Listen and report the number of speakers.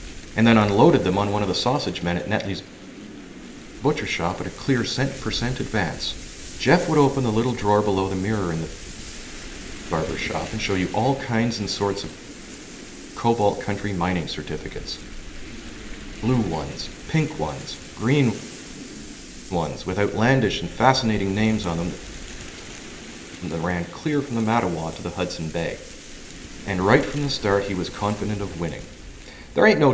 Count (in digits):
1